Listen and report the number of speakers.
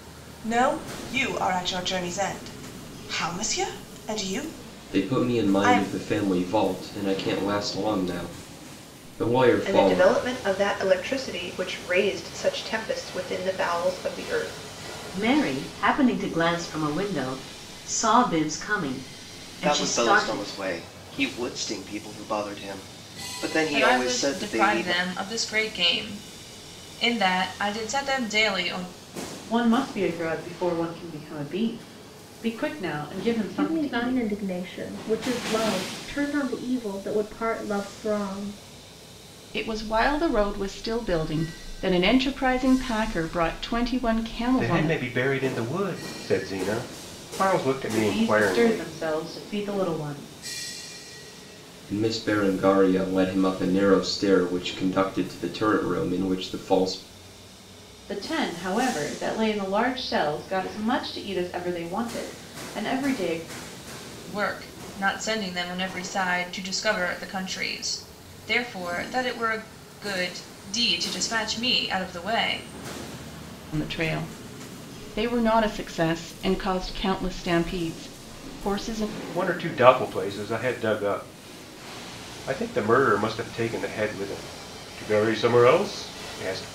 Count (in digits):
10